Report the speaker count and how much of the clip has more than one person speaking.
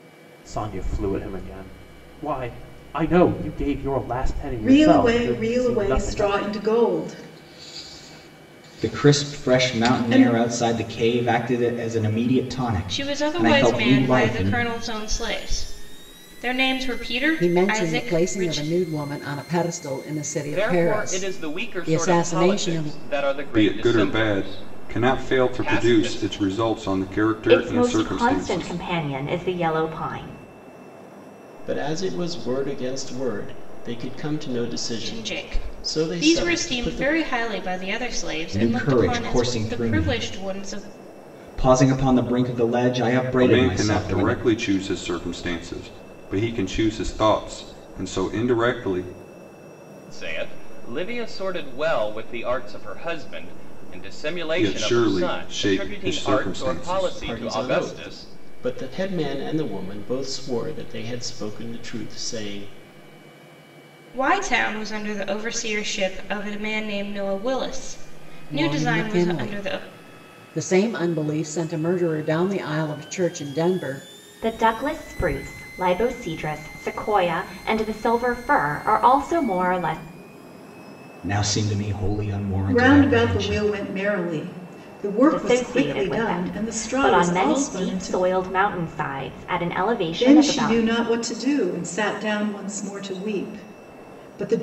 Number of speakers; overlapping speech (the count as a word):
nine, about 30%